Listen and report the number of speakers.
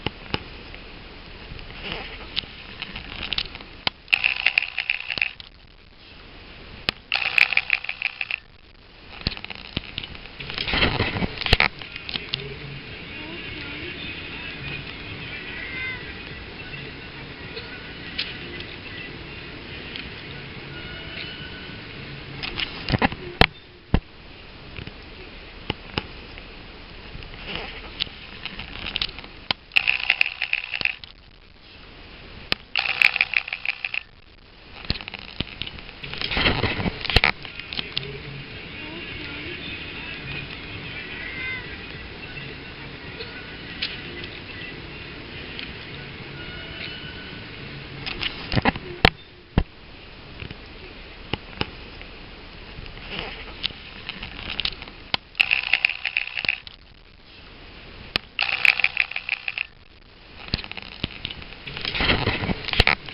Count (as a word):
zero